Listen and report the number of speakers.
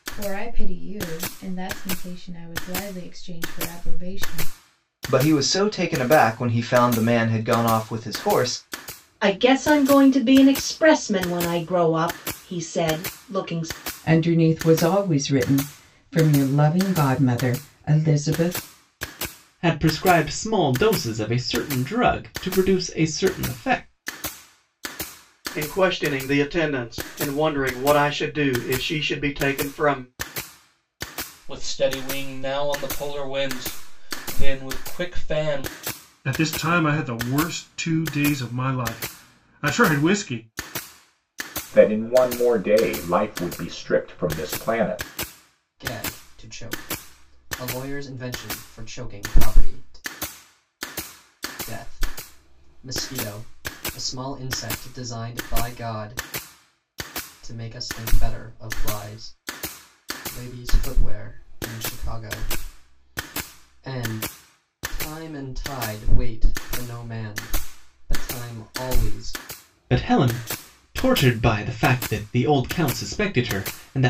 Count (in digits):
10